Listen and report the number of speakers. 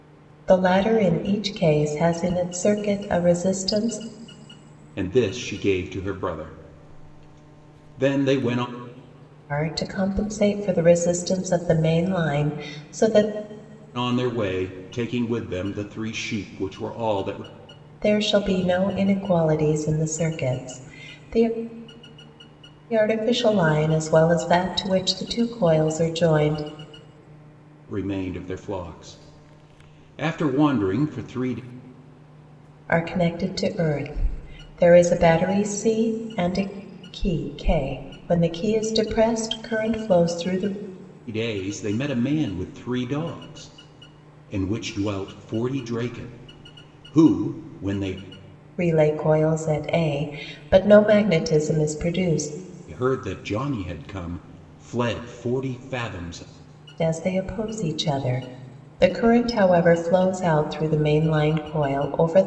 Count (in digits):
2